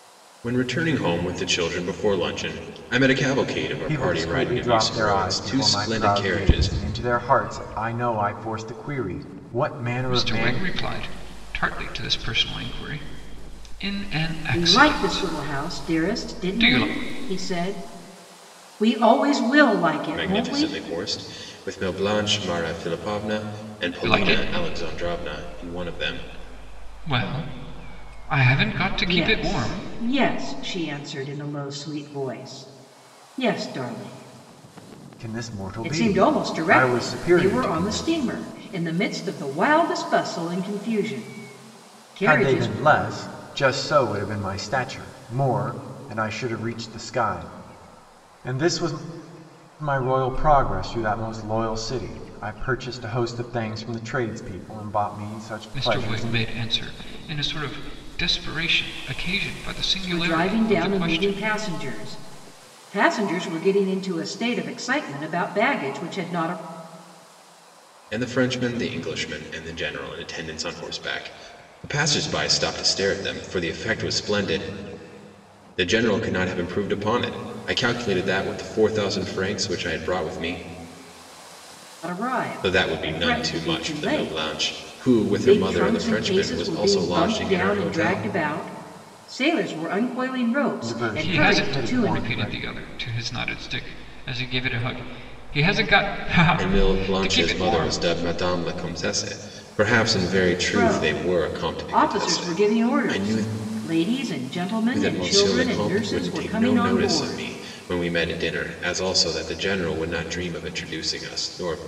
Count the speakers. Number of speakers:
4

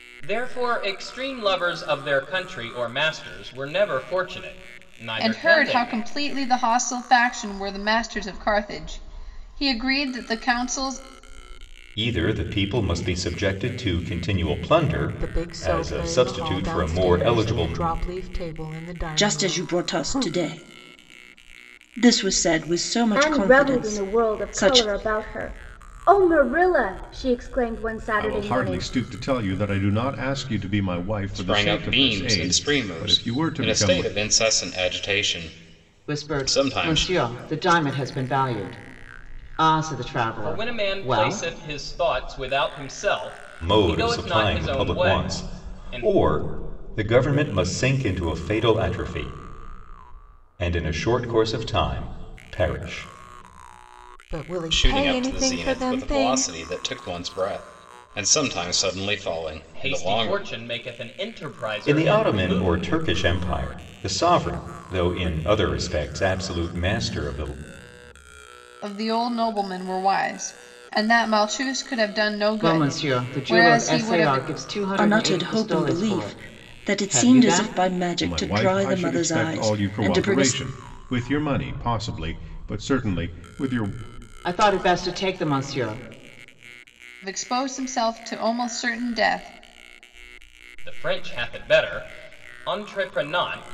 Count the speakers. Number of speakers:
9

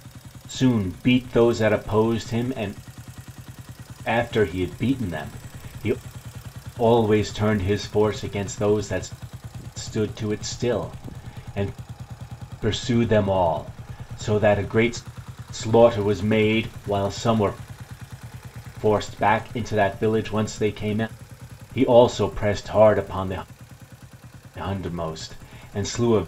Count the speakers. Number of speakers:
1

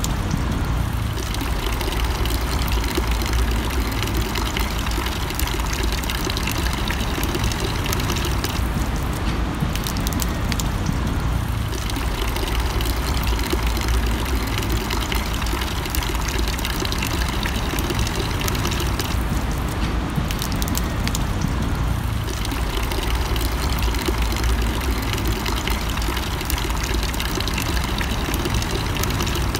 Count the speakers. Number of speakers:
0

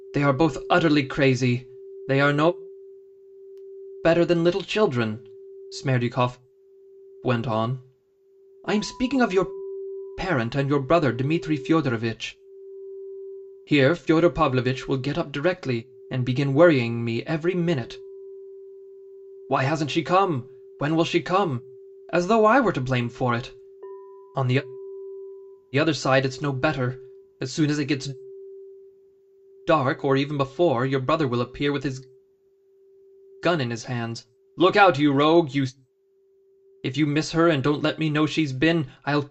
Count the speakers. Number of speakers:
1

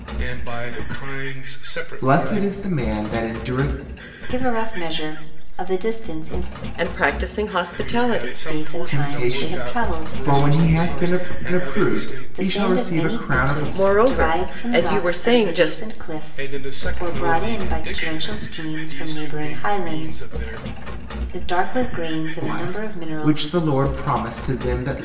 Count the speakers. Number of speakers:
4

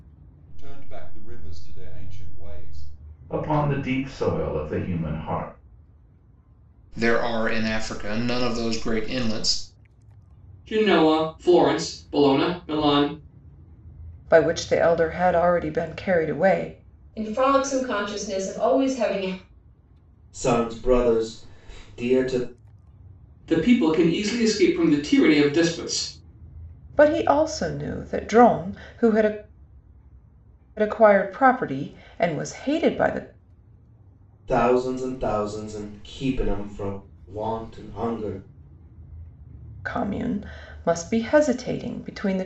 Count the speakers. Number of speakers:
7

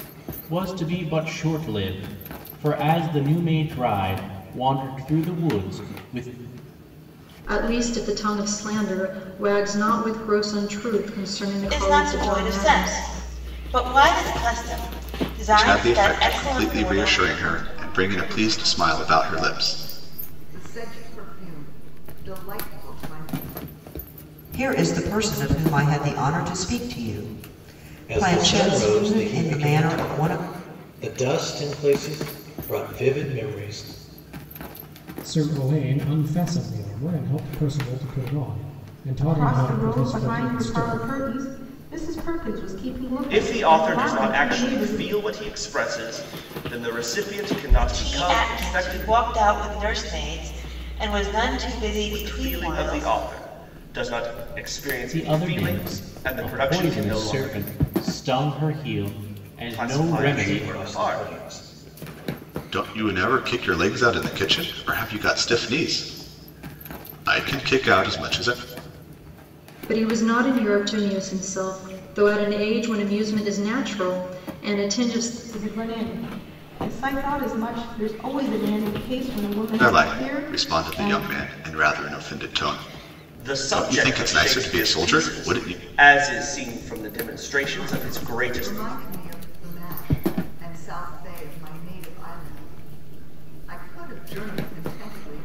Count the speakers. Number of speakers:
10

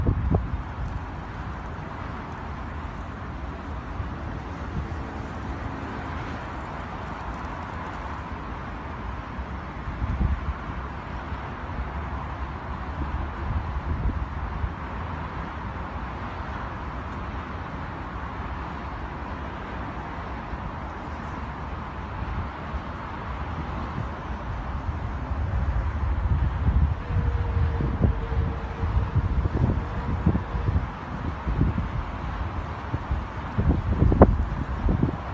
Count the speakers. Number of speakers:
0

